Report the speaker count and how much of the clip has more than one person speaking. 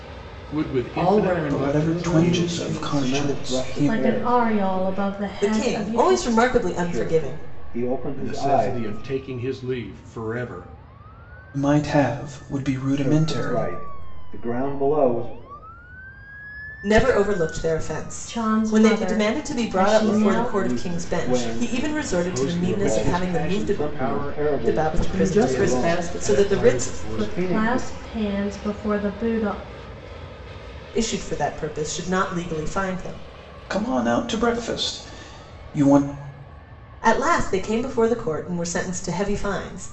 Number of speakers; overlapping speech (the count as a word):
six, about 43%